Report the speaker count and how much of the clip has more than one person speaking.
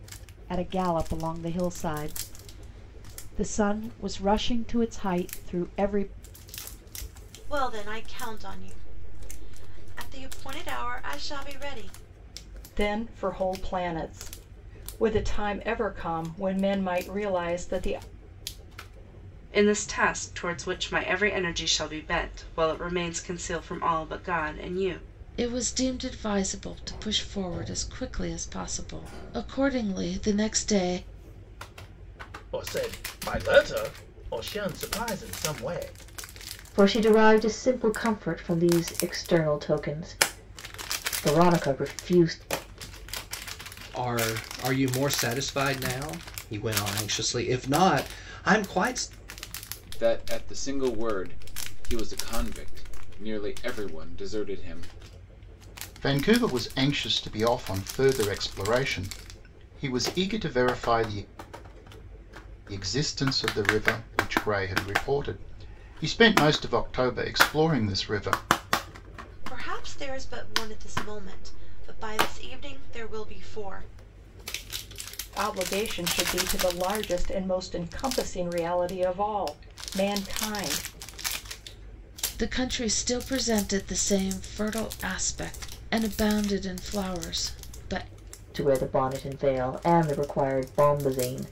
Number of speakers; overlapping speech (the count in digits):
10, no overlap